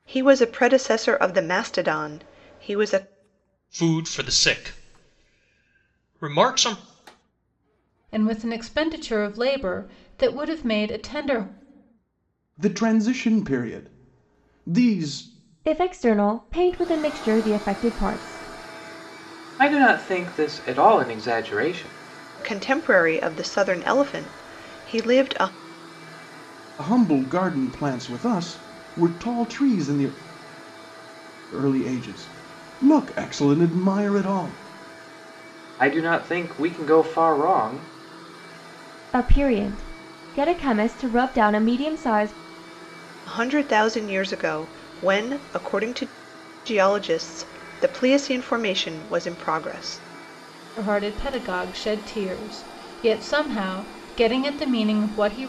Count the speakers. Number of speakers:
six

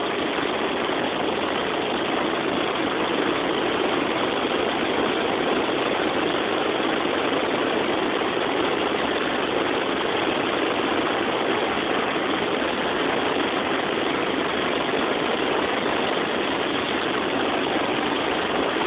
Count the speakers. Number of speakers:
zero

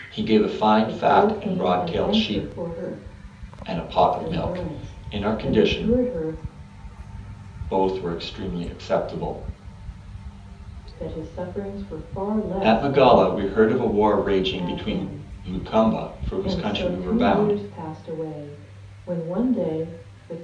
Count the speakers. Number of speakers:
two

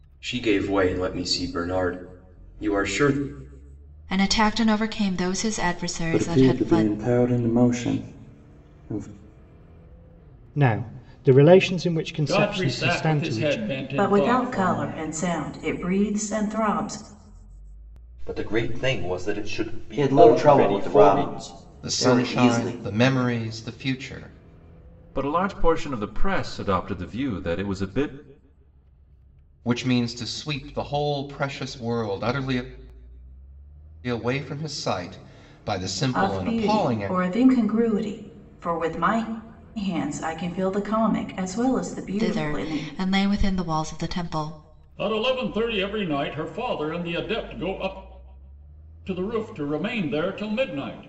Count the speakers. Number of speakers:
ten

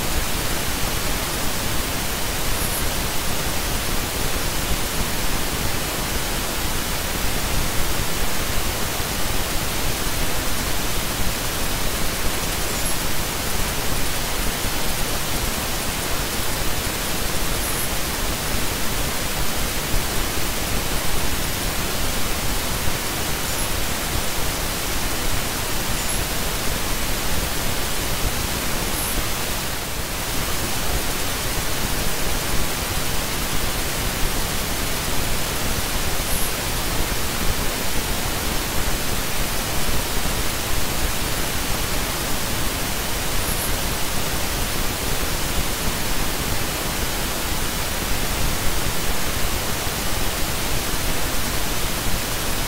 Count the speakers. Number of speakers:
zero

